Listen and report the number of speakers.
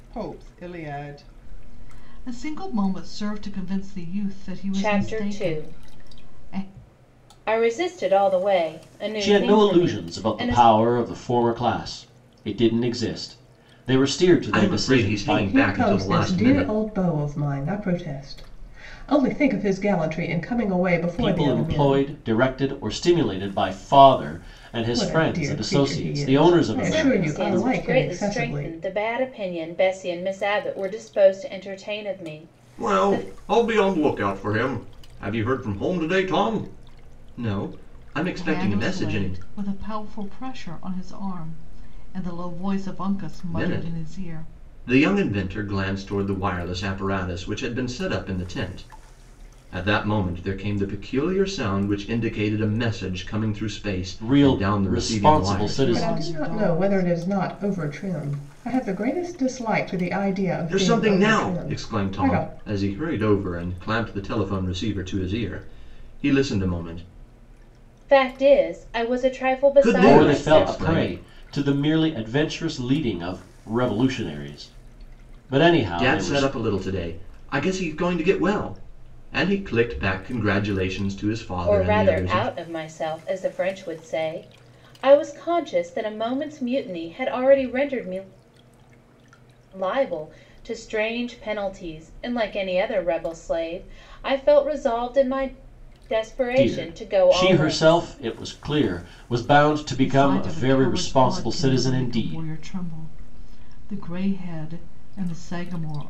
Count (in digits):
5